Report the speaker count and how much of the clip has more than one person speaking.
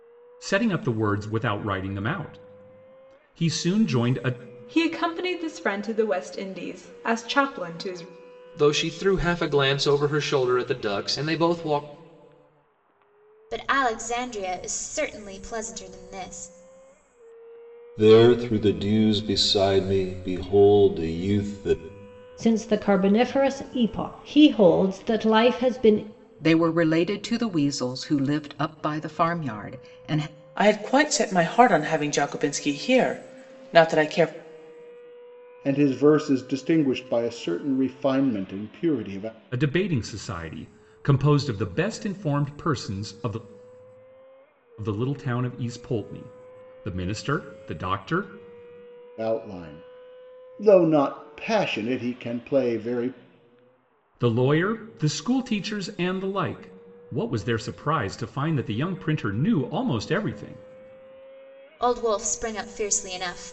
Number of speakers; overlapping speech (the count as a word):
nine, no overlap